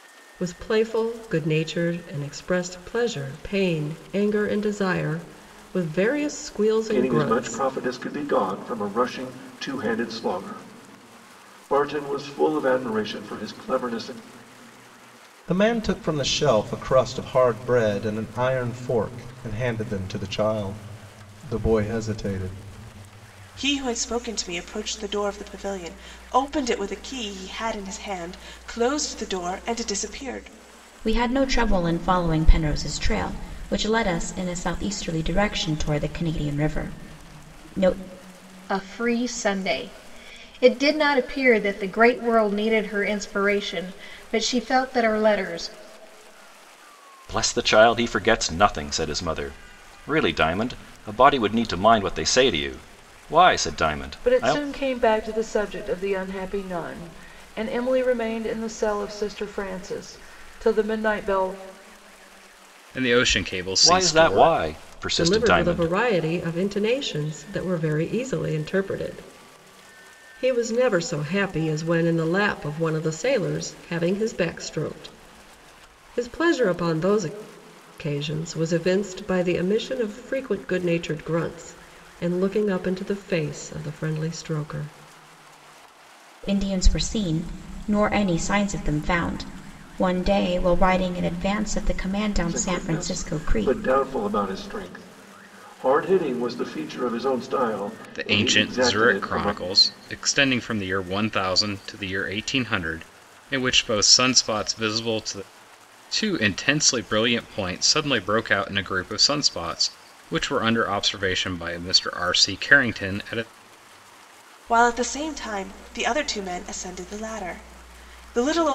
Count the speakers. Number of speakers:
9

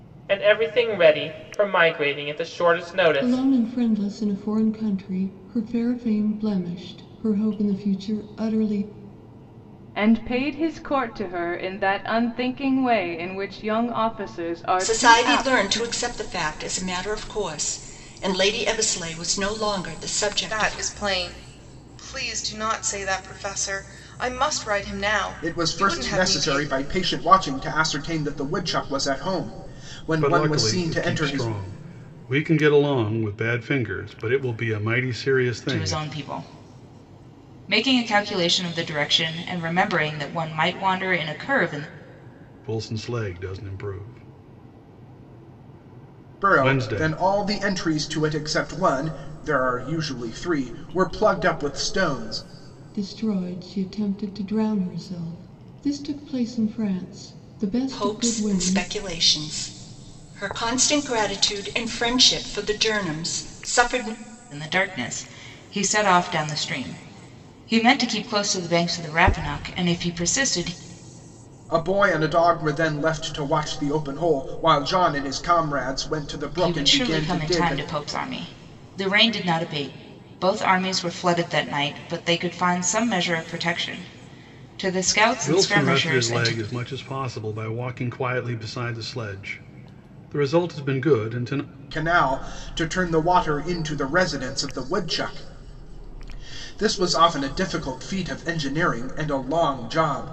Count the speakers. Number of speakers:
8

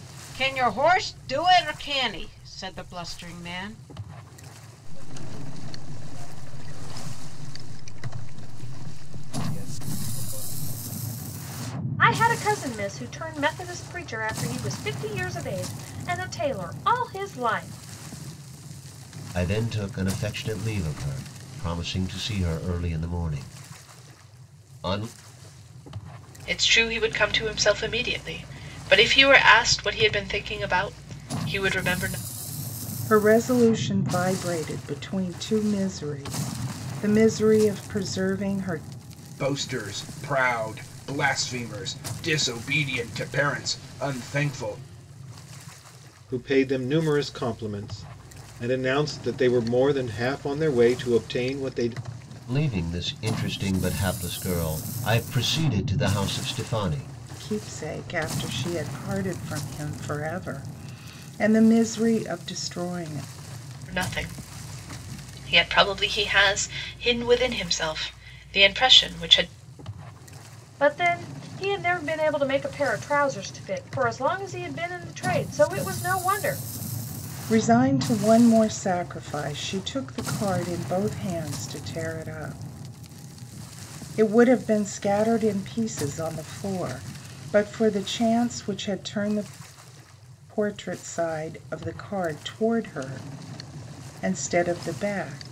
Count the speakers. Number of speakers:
8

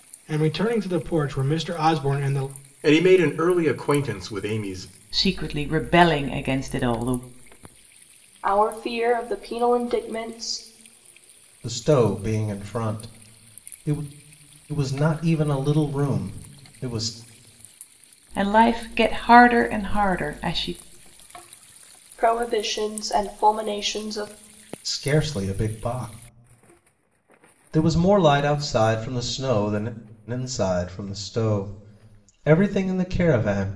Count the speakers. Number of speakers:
5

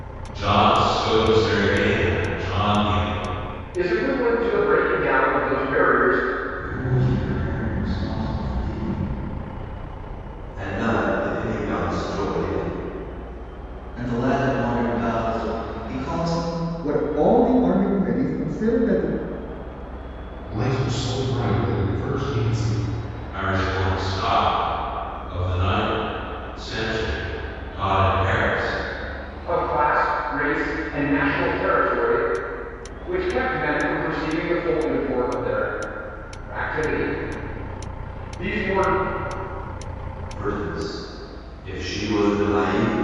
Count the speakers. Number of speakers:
7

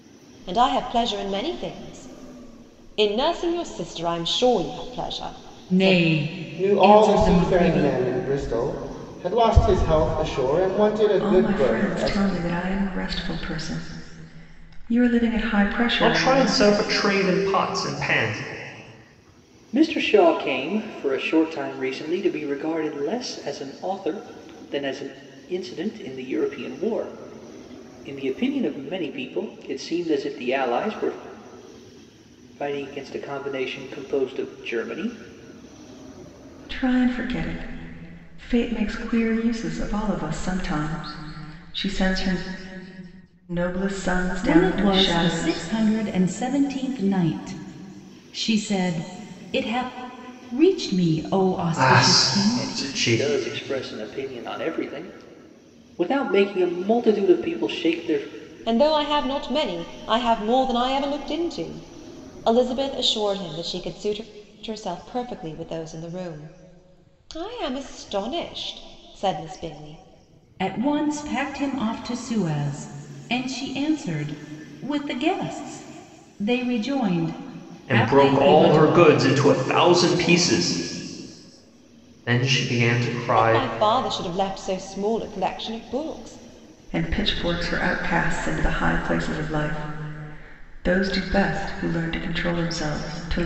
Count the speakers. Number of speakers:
6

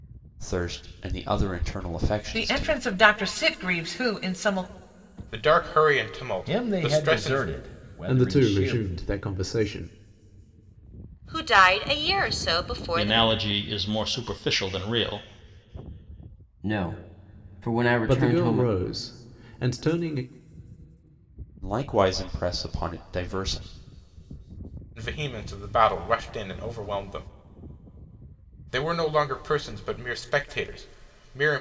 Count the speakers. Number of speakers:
8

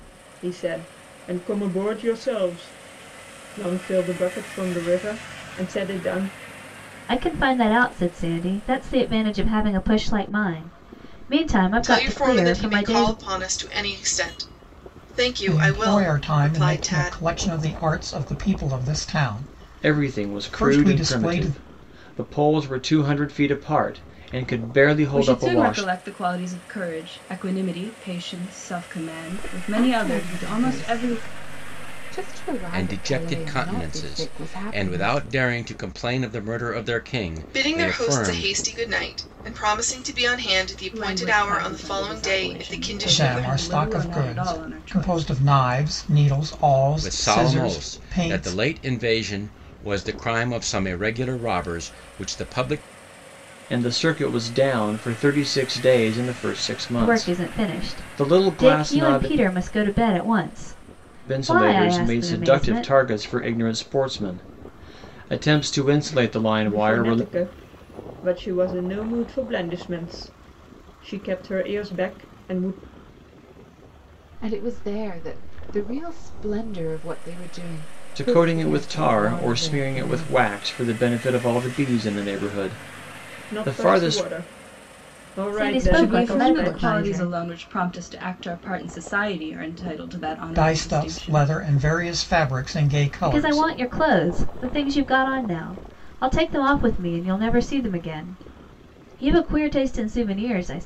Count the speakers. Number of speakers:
8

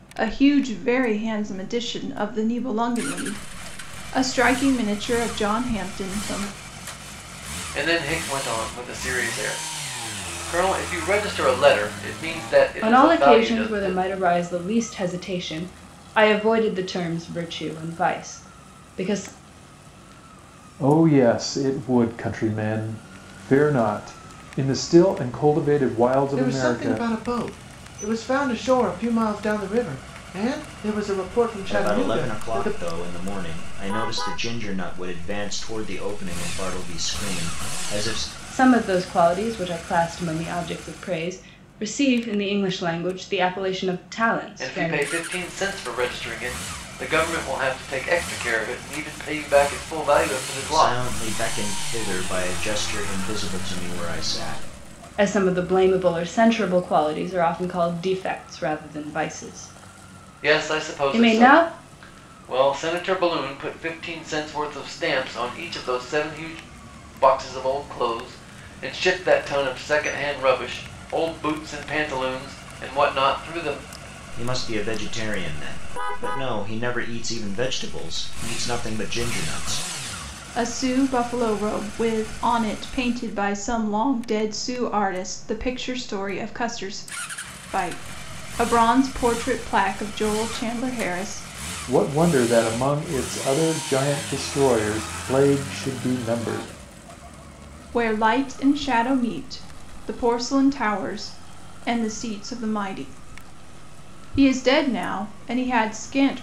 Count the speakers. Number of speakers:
6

